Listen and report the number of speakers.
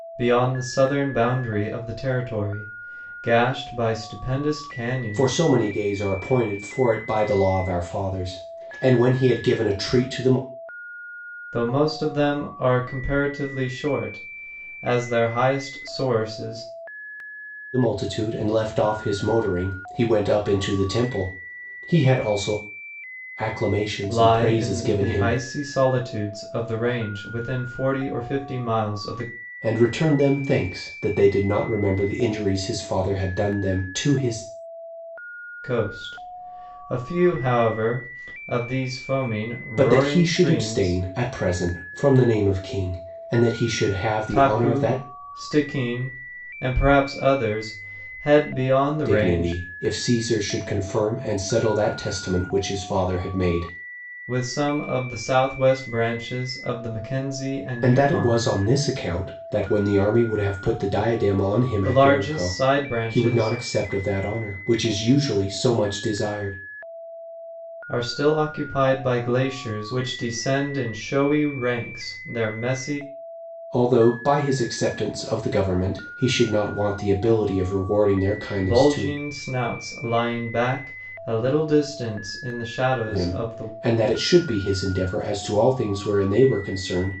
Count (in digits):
2